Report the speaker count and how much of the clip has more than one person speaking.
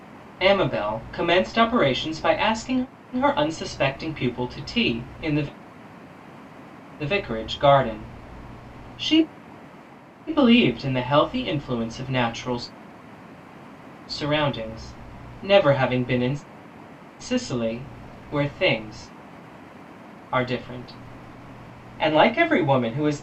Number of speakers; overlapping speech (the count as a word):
one, no overlap